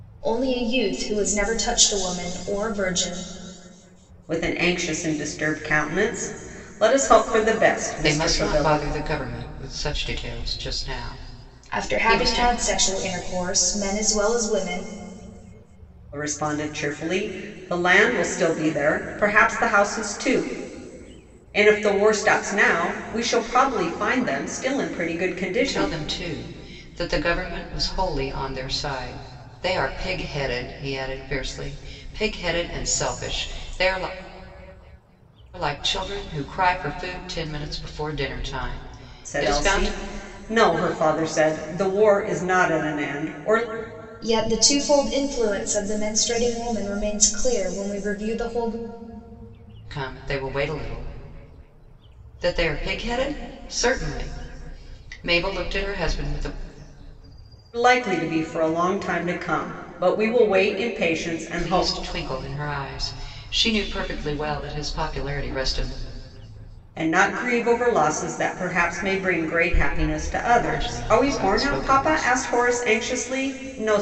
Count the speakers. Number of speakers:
three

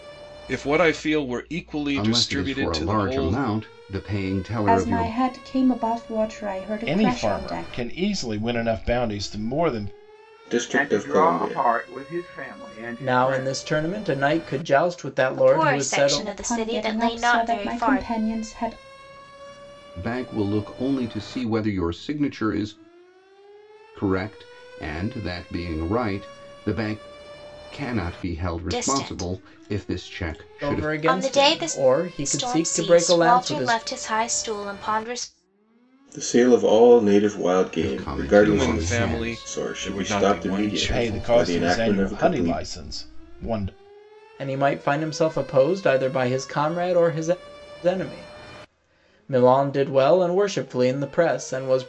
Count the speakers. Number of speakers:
eight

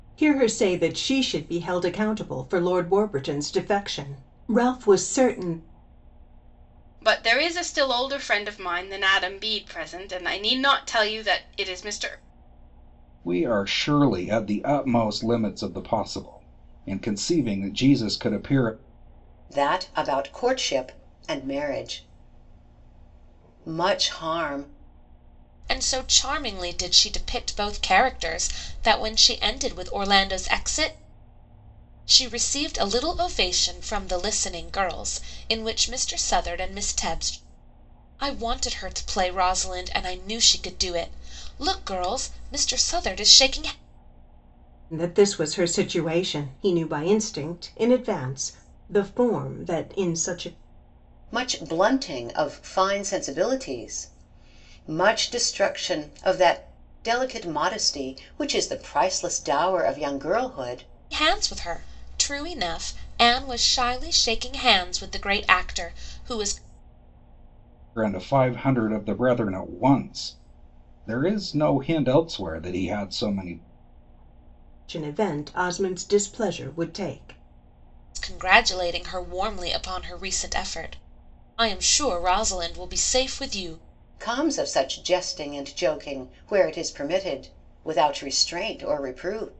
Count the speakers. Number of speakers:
five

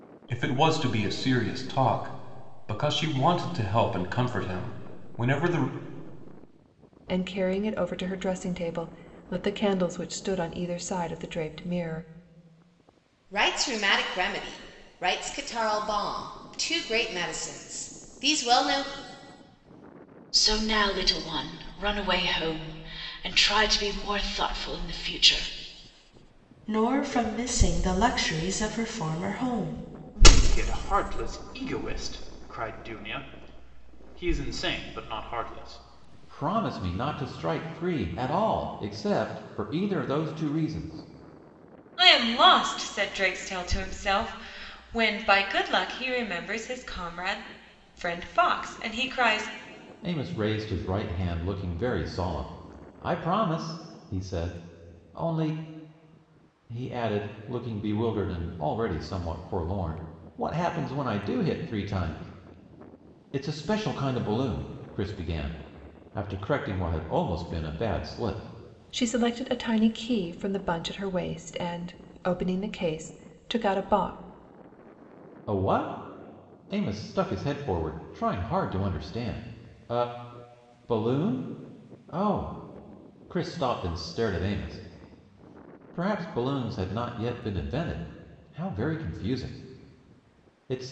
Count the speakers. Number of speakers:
eight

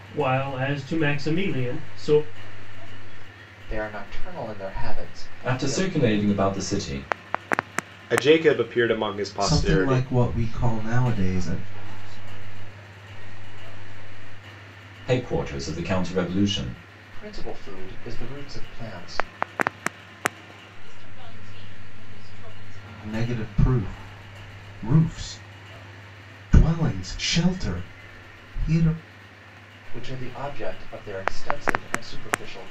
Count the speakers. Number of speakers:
seven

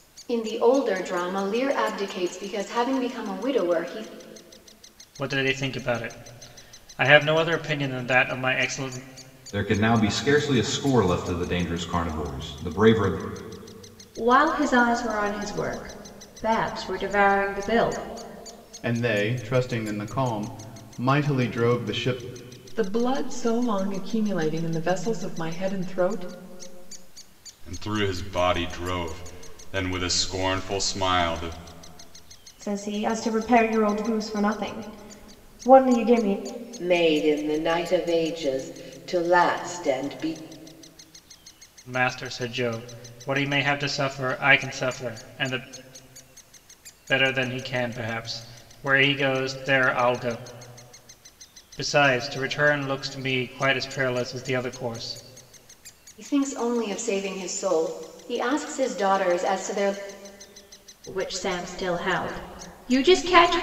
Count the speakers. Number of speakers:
nine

